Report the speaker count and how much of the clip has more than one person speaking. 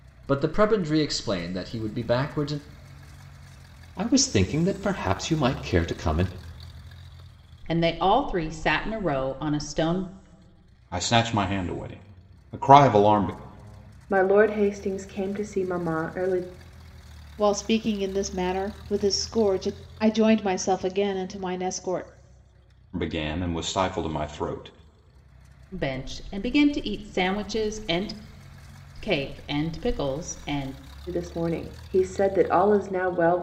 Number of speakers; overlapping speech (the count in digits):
6, no overlap